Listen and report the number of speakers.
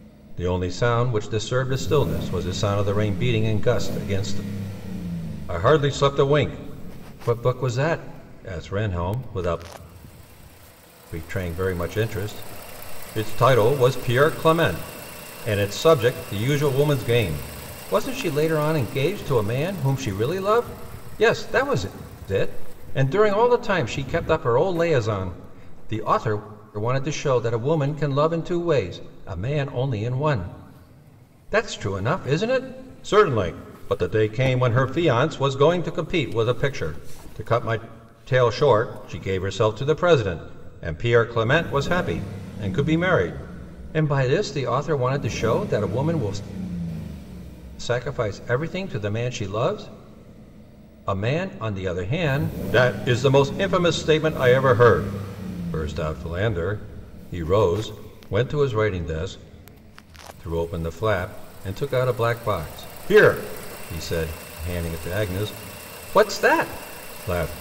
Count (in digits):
1